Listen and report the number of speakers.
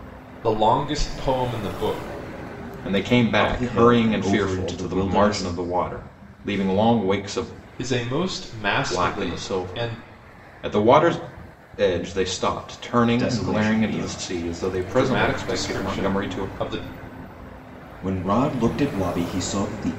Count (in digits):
3